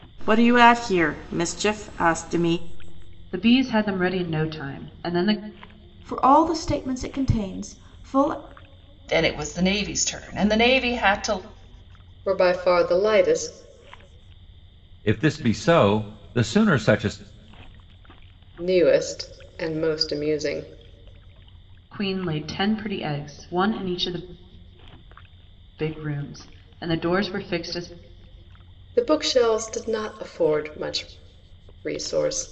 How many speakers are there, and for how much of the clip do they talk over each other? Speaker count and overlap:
six, no overlap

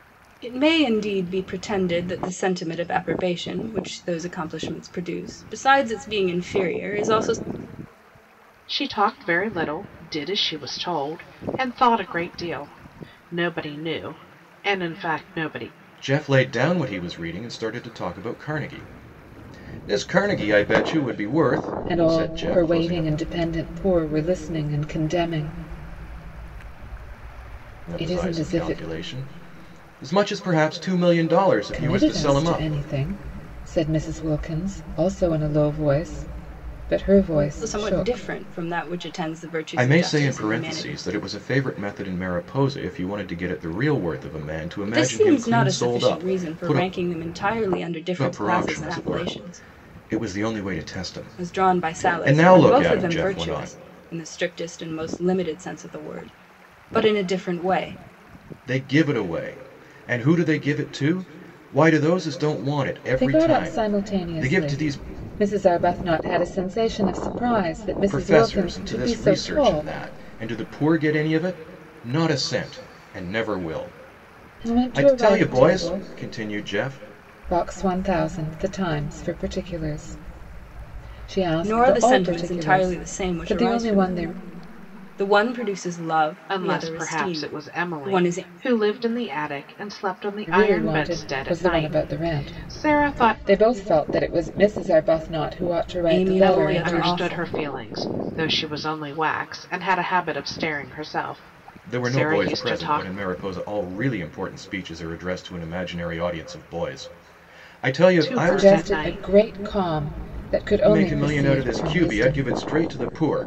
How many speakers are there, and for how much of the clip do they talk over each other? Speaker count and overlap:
four, about 26%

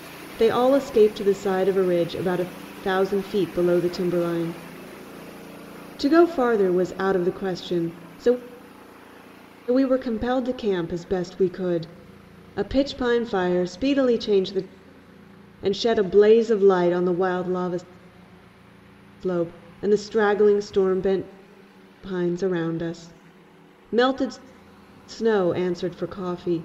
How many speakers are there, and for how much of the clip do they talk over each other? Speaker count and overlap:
one, no overlap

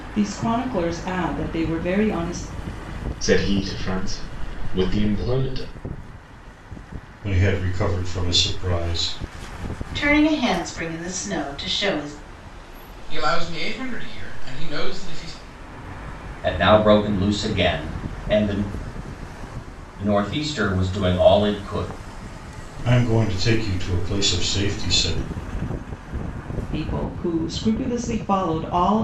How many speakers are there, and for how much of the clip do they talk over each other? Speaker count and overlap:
six, no overlap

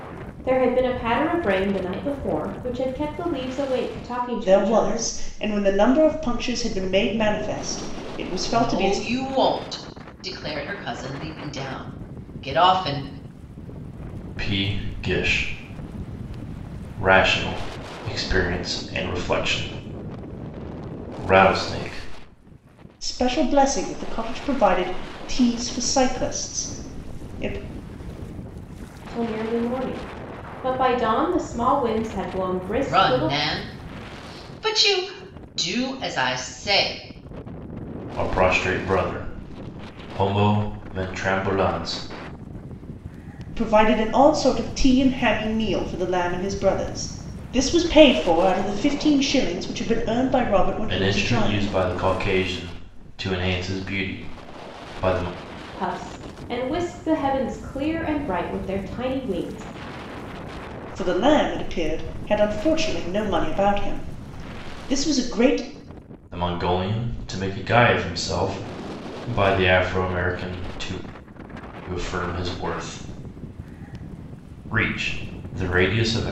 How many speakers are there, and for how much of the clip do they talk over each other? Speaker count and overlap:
four, about 3%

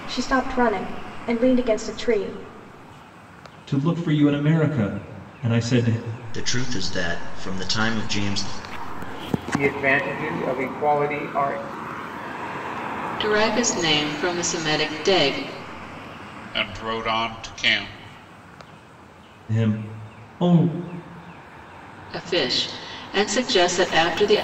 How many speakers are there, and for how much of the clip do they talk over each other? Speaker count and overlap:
six, no overlap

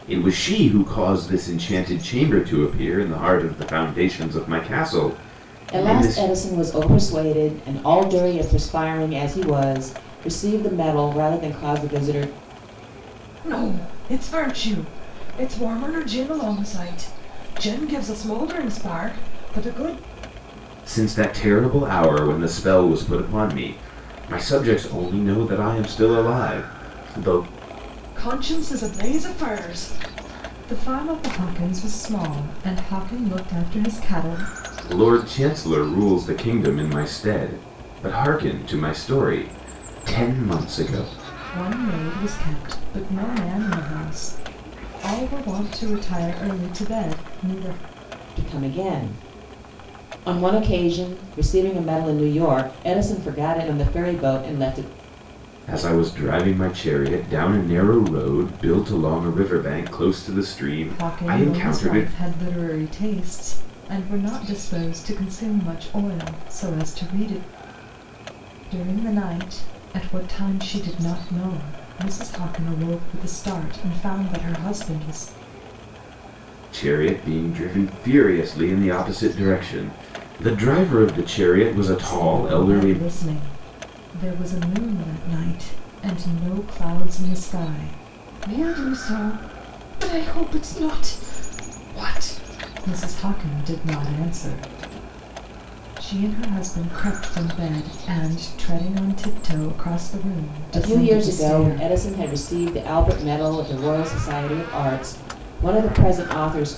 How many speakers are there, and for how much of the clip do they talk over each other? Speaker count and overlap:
three, about 4%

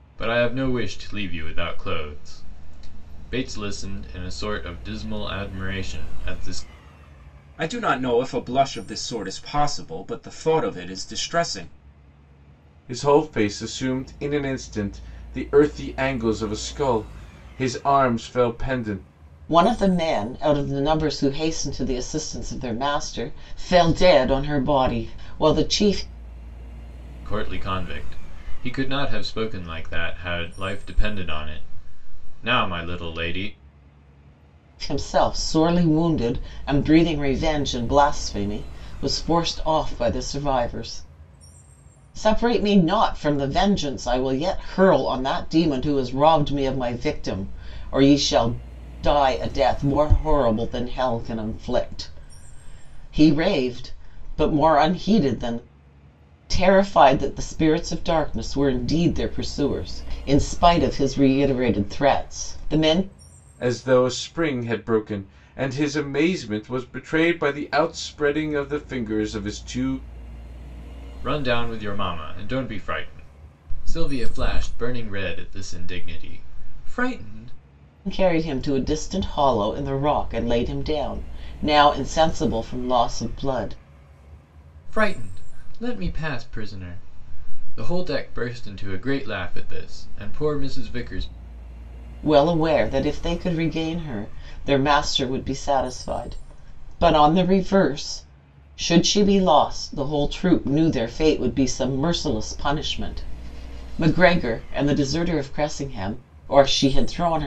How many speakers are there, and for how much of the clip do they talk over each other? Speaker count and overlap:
four, no overlap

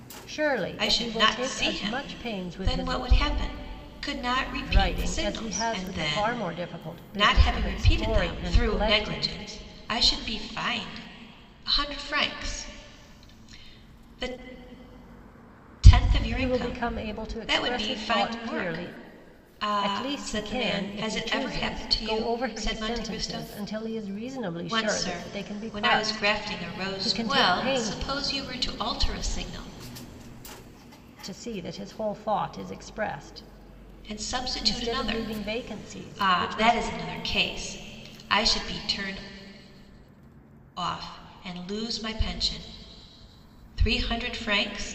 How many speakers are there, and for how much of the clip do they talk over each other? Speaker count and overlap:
two, about 42%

